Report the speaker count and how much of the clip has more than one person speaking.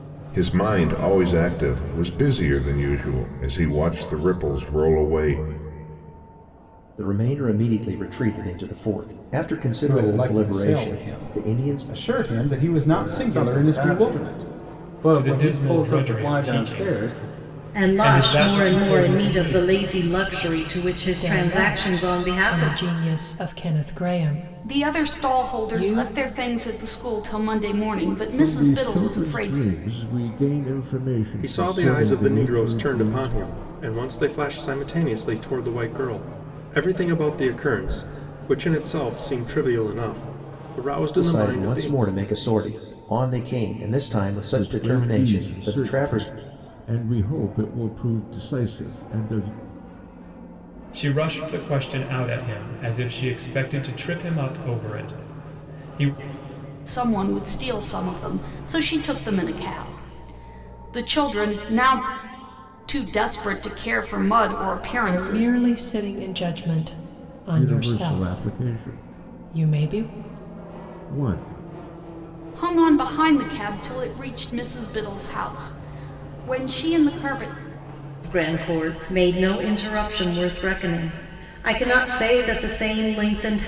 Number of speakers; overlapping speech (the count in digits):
10, about 24%